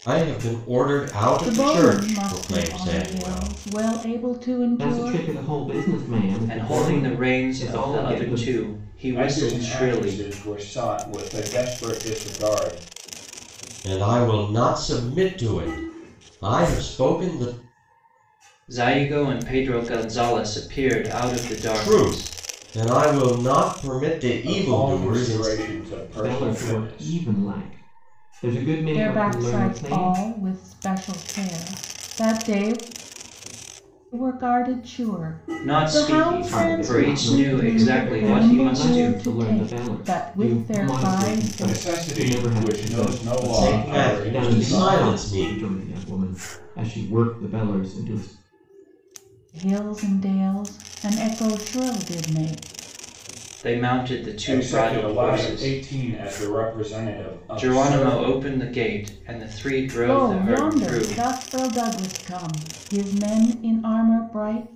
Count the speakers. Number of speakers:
five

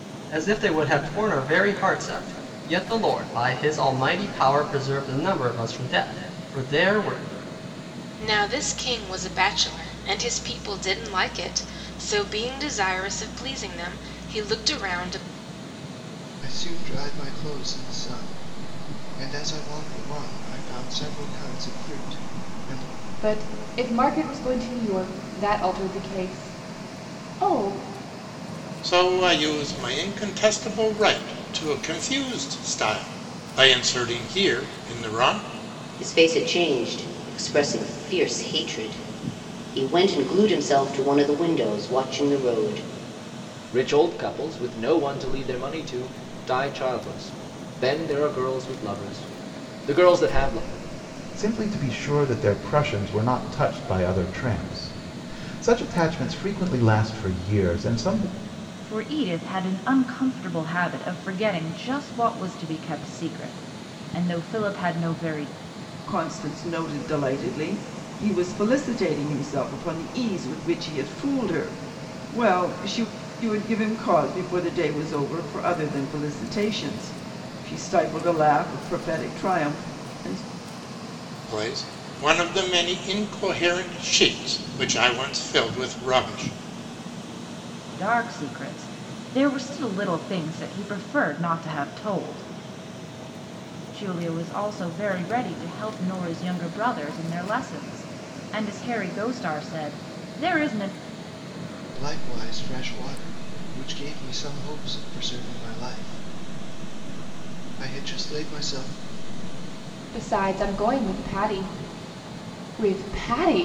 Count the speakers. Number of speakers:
ten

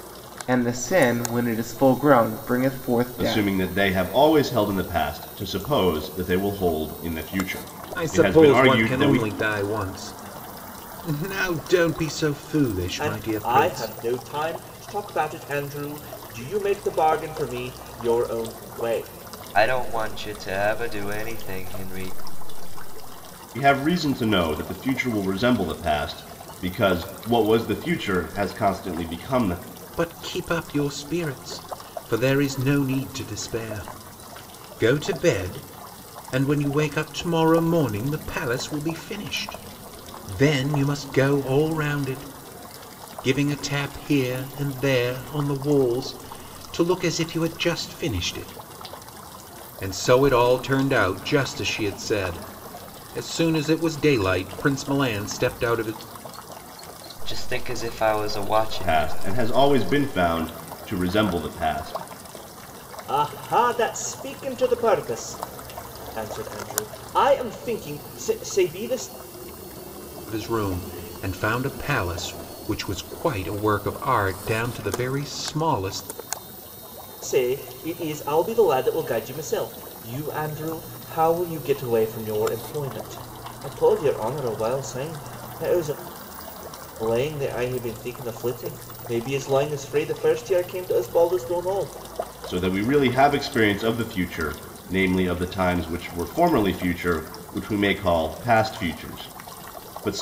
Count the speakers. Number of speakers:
five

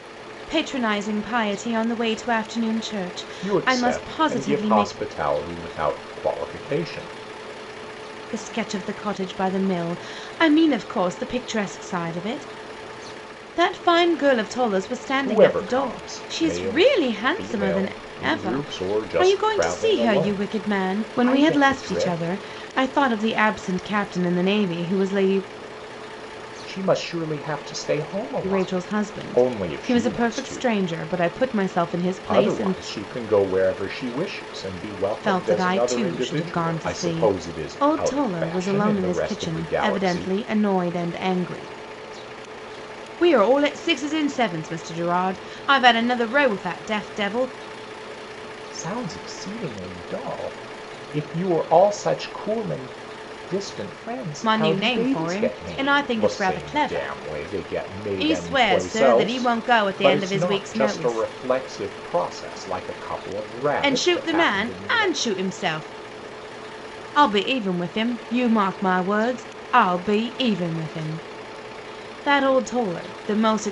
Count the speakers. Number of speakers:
two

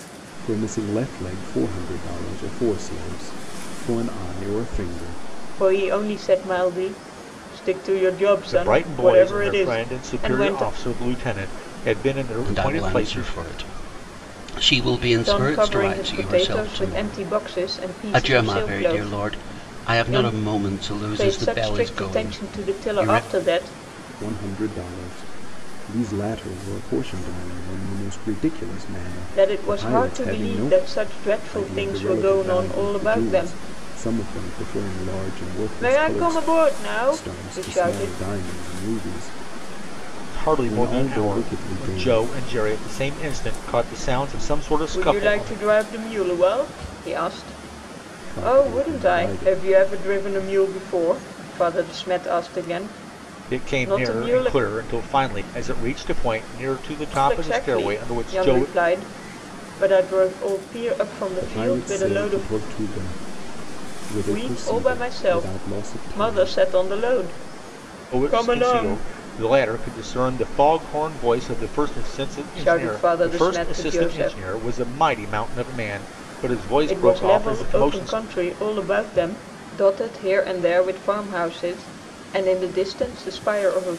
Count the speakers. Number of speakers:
four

